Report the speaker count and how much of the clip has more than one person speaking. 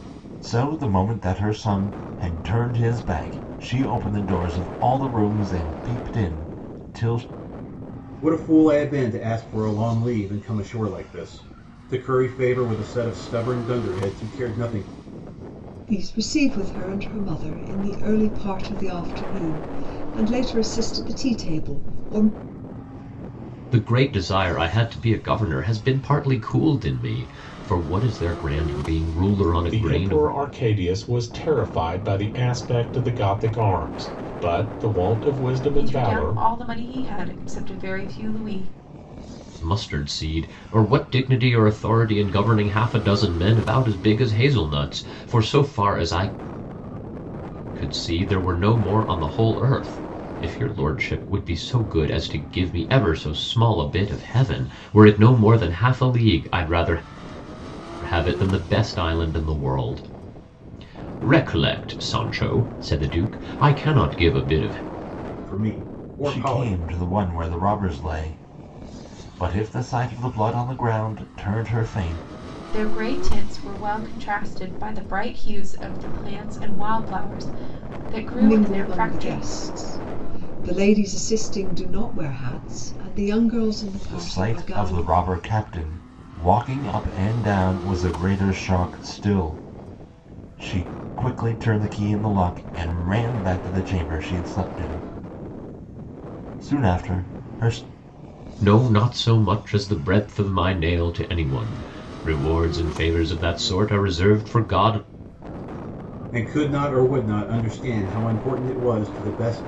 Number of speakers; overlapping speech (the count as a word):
six, about 4%